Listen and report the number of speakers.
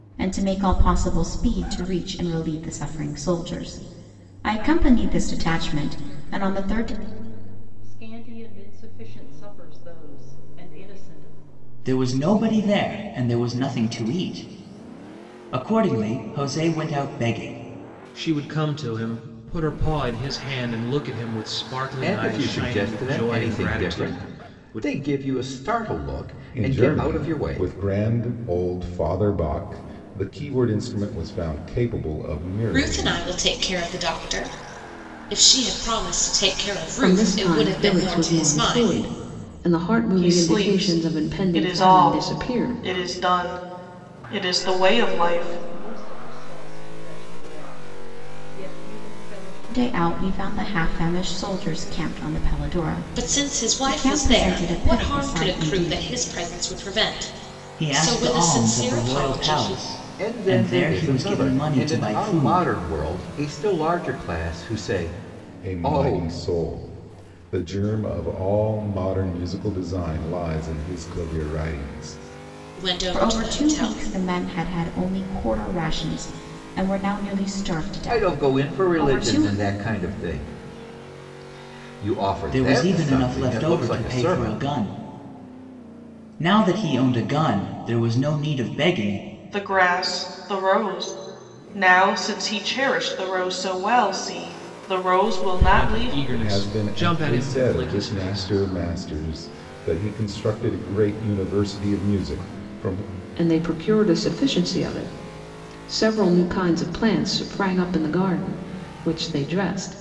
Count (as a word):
nine